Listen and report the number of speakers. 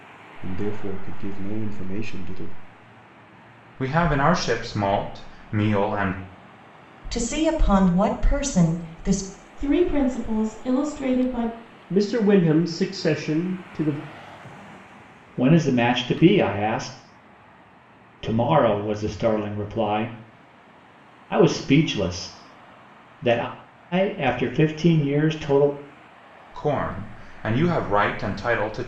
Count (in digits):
6